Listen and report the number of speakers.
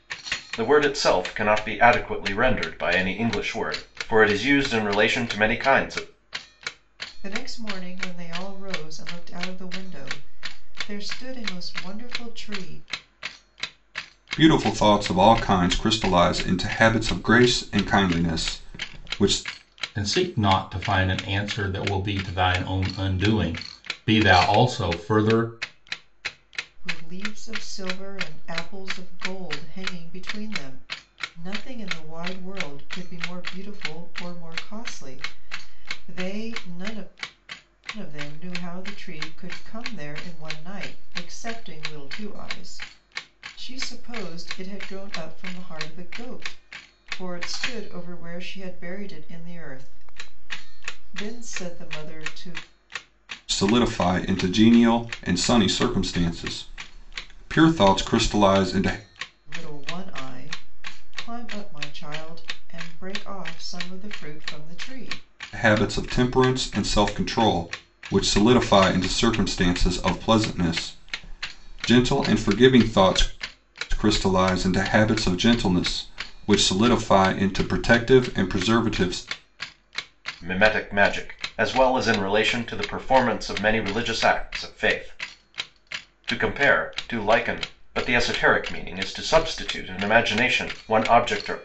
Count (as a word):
four